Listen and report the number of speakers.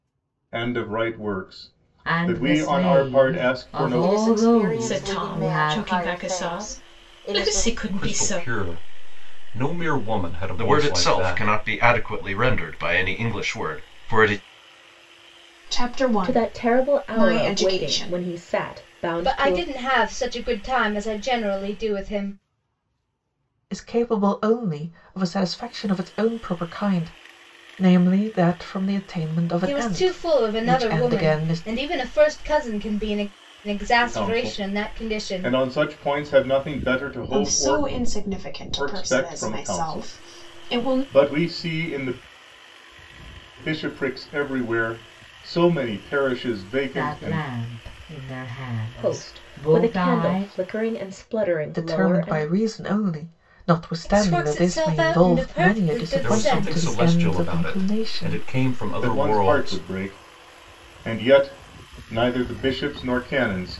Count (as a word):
ten